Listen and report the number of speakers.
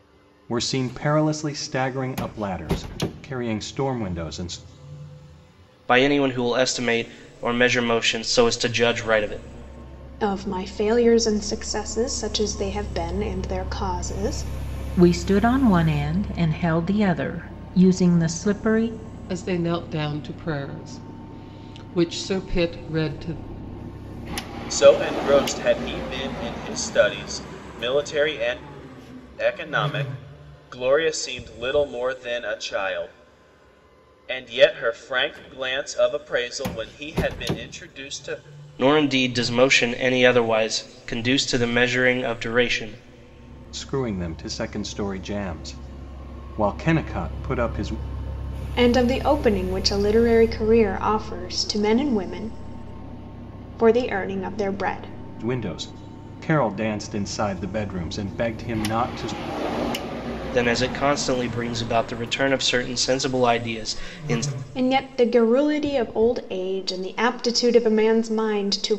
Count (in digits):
6